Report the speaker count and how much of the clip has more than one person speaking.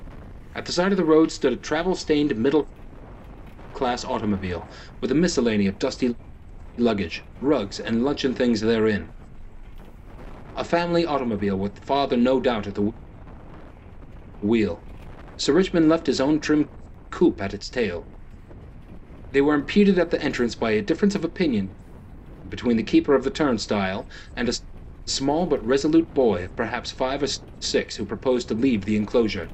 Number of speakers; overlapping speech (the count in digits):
1, no overlap